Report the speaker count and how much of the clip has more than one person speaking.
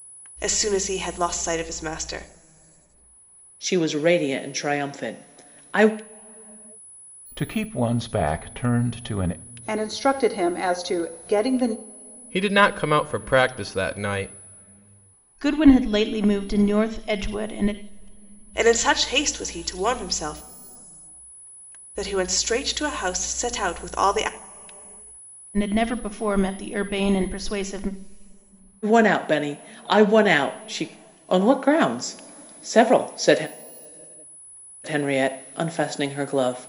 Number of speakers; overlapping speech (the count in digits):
6, no overlap